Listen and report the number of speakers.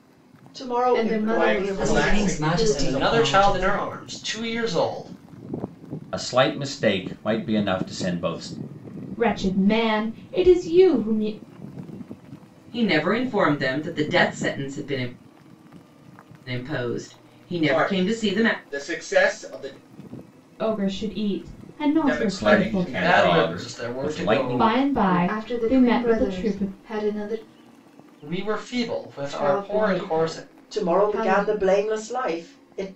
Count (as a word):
eight